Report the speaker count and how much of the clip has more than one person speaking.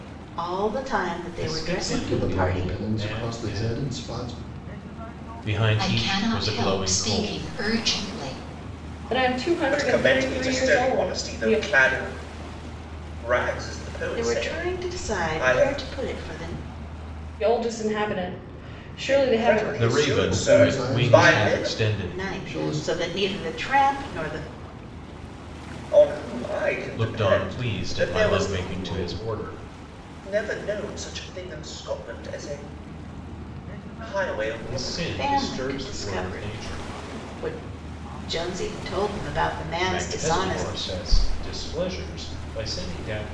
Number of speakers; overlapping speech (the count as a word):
seven, about 41%